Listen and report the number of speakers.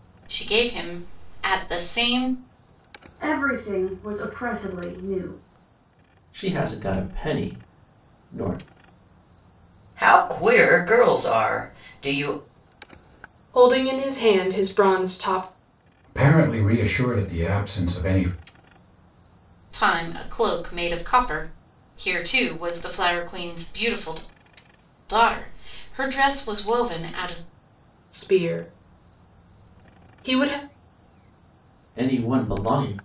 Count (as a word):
six